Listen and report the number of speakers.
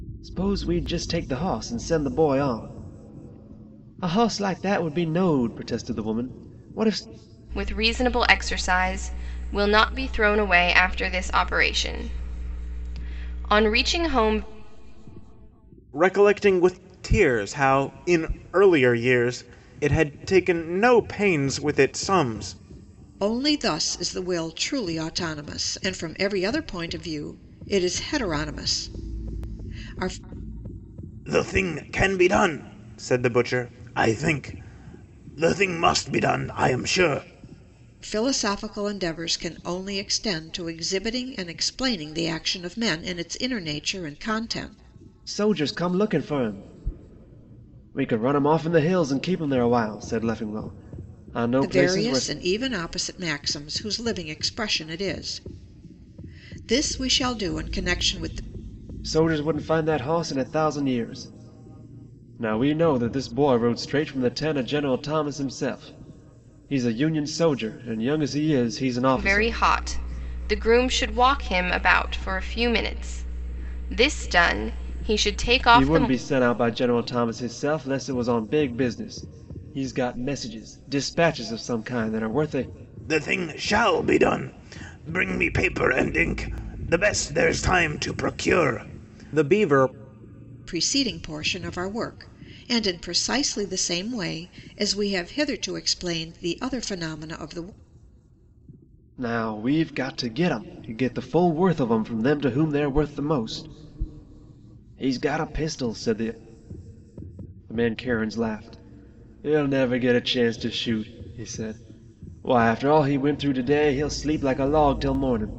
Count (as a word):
four